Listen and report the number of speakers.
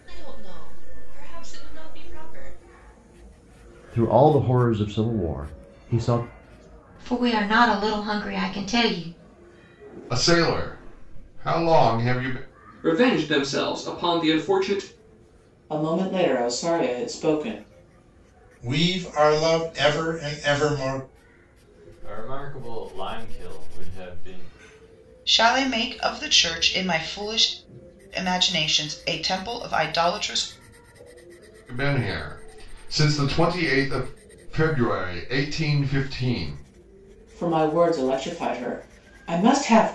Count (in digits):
9